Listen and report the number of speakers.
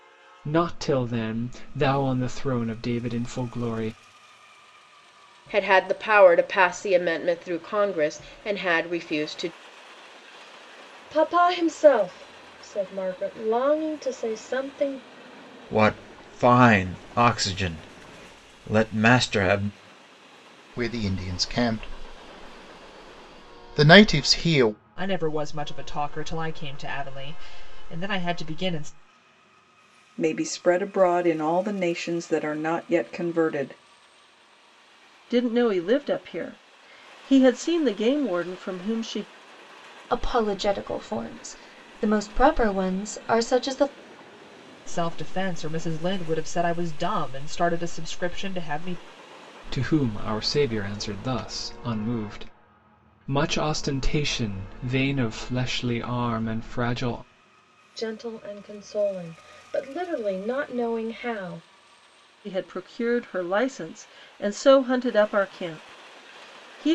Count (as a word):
nine